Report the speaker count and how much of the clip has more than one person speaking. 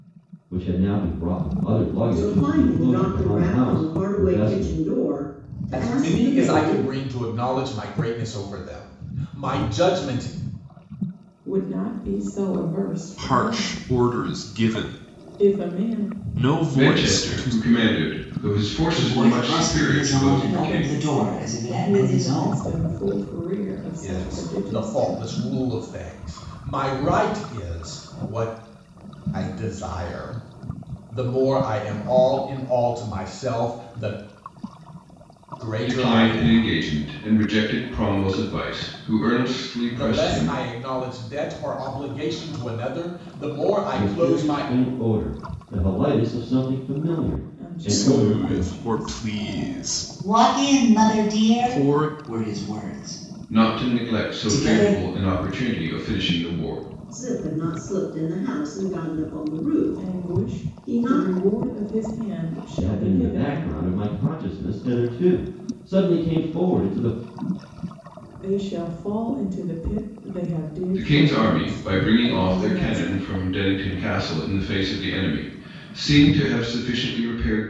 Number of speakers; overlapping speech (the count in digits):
7, about 32%